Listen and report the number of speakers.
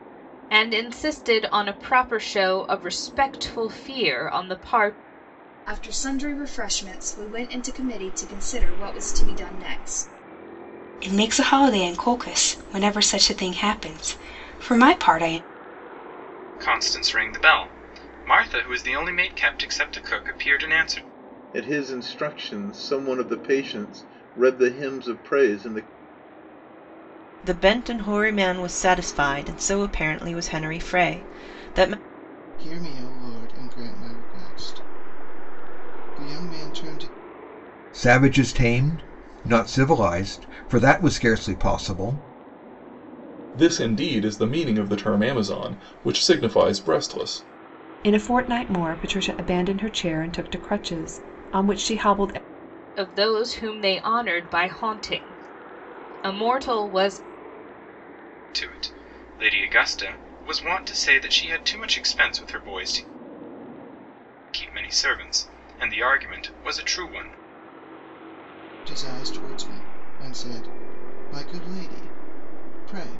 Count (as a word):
ten